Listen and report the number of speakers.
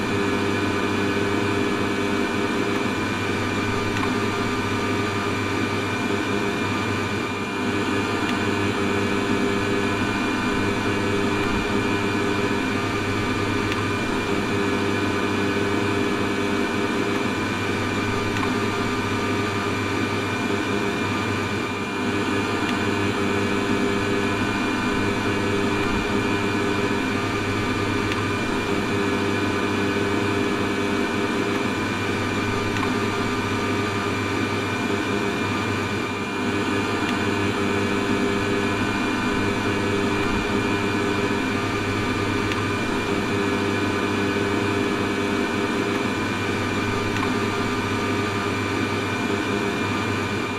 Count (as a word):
zero